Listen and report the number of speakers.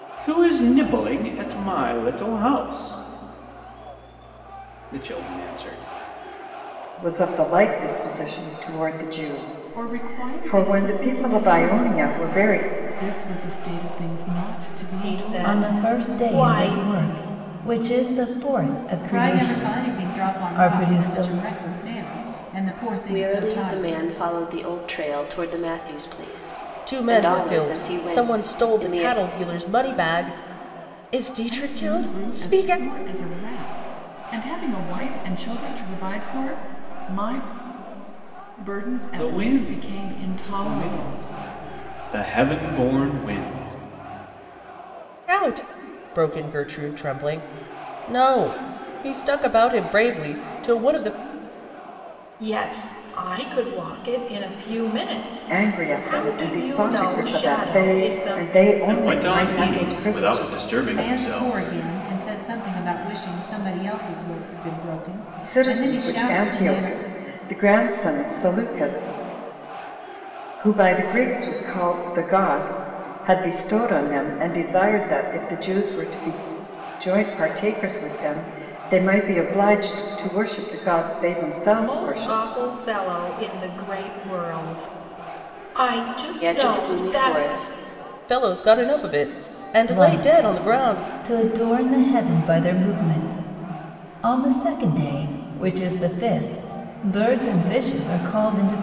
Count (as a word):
eight